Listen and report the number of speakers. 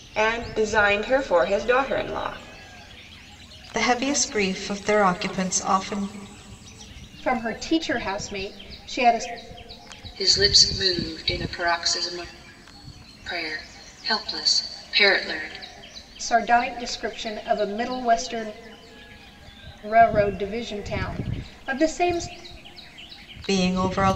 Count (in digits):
4